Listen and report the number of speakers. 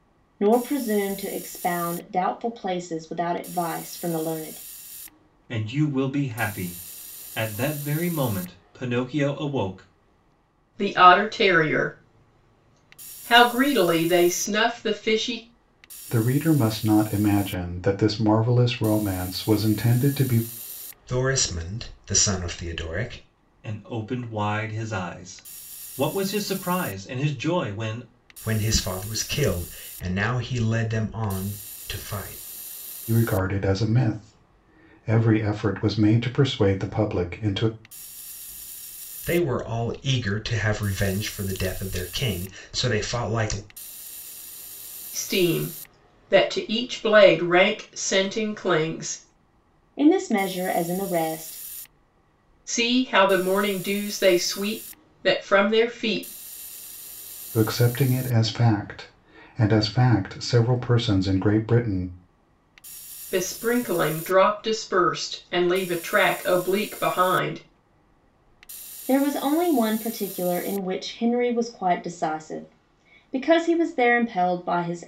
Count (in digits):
5